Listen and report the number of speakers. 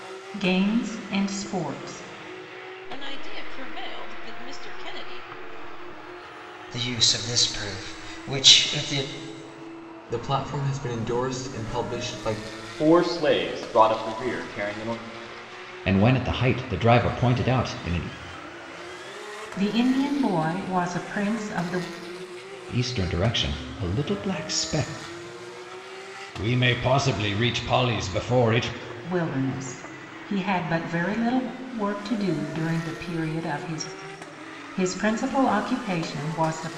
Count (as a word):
six